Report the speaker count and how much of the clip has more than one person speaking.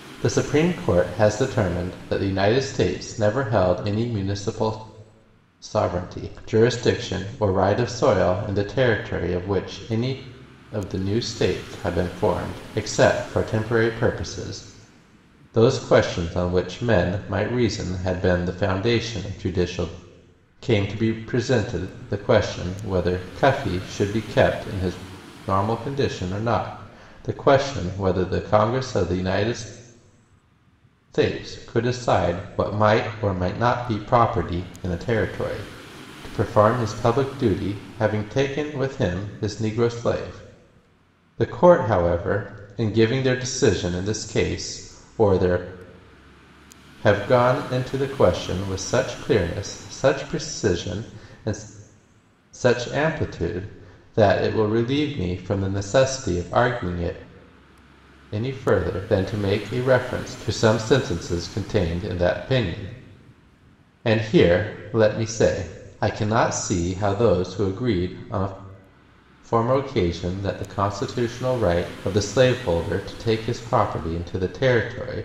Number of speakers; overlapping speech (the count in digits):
1, no overlap